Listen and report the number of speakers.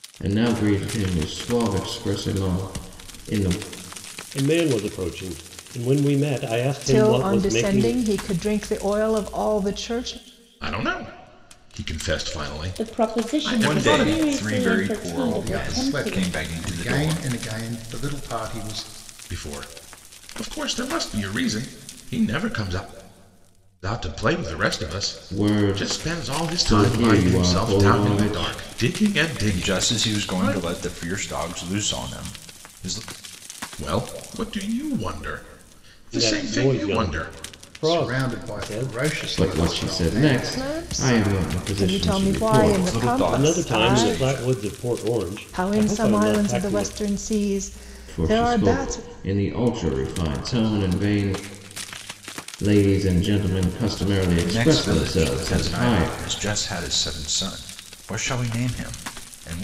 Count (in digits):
7